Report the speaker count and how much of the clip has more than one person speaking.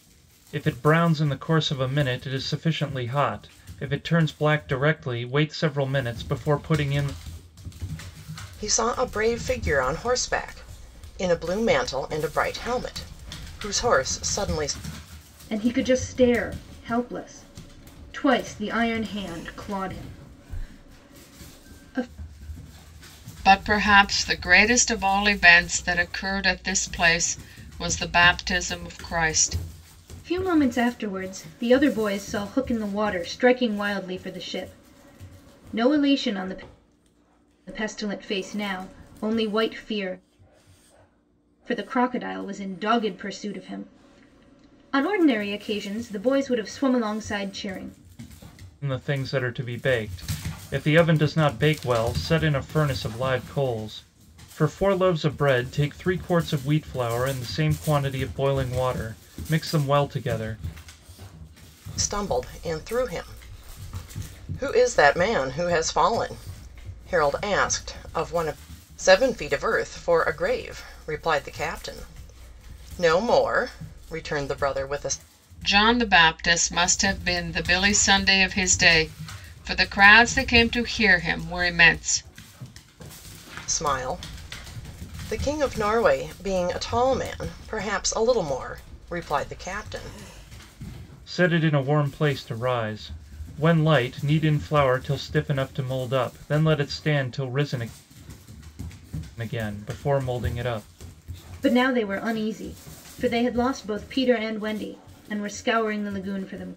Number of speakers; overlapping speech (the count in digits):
4, no overlap